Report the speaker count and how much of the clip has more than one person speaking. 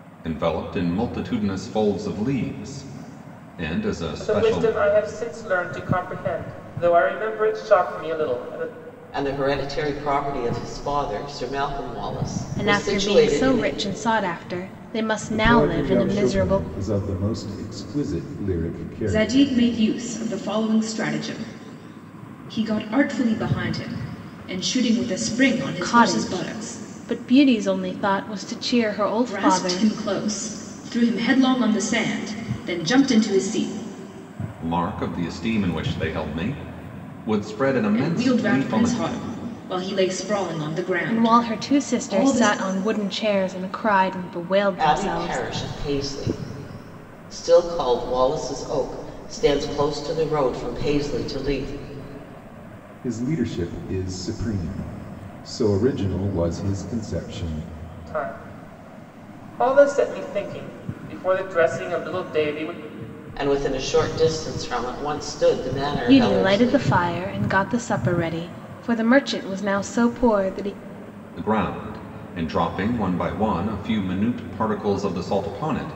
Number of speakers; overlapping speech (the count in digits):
6, about 13%